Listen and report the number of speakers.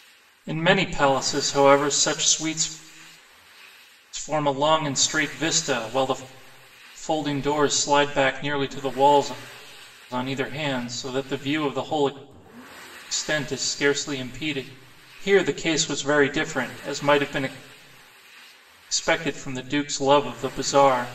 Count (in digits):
1